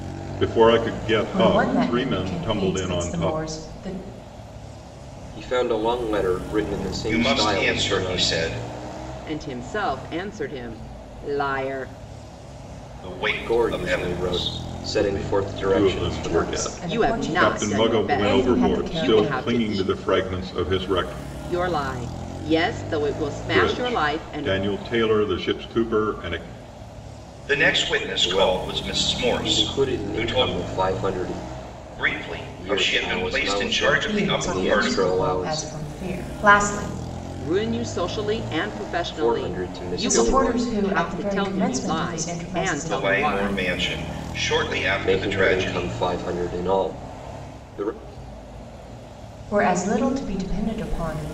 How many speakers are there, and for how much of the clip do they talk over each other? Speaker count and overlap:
5, about 42%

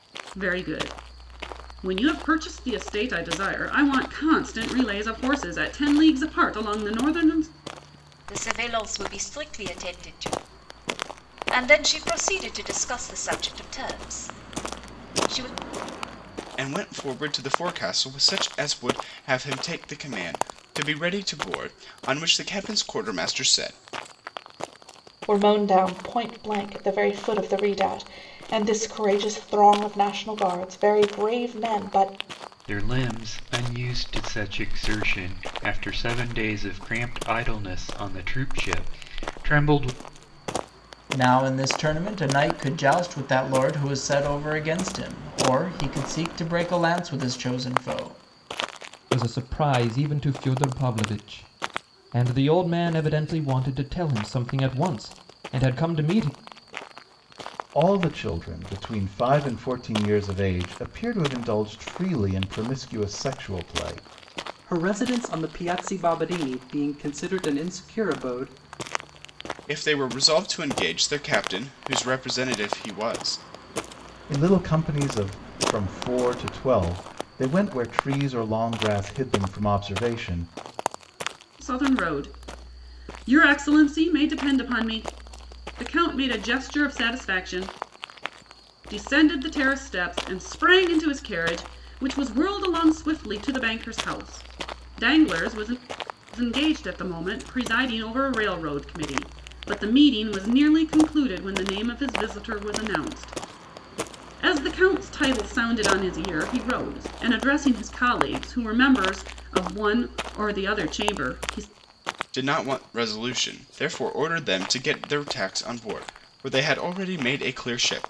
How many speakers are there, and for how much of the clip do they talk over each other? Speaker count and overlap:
9, no overlap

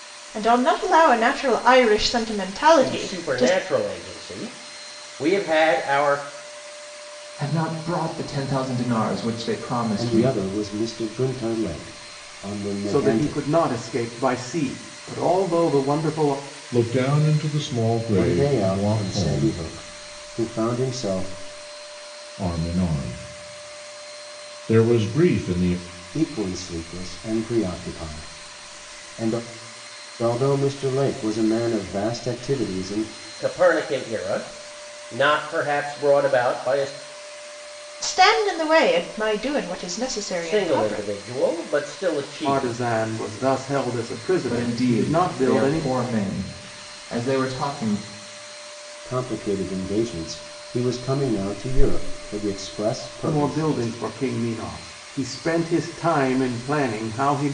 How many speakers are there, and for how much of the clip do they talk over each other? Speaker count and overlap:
6, about 11%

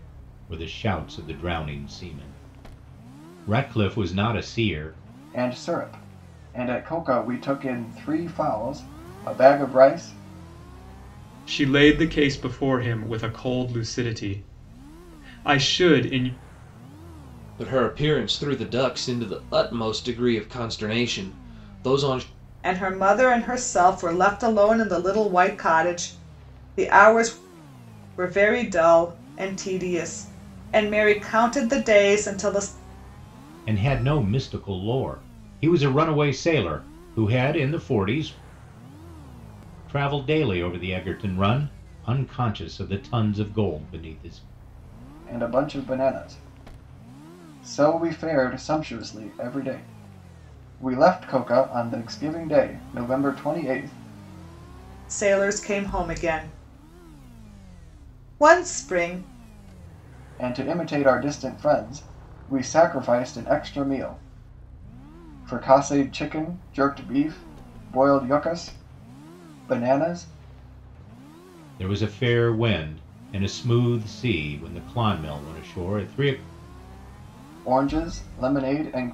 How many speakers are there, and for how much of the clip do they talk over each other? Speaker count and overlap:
5, no overlap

